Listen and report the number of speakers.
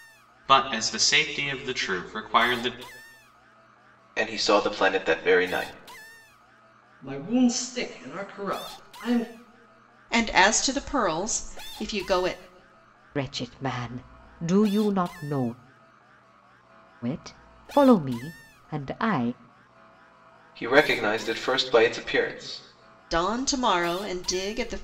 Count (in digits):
5